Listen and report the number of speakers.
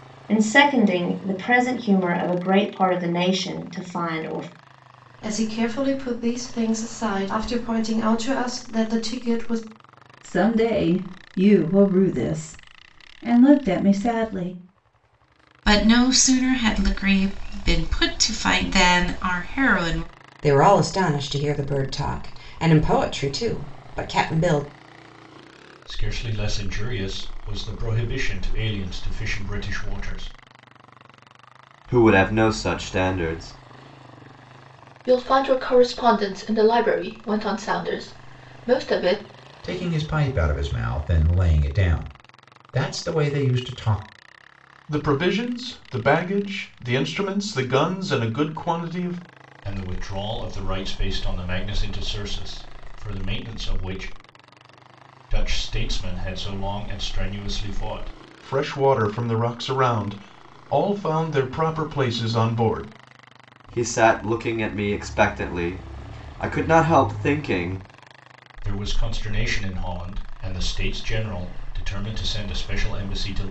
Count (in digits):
10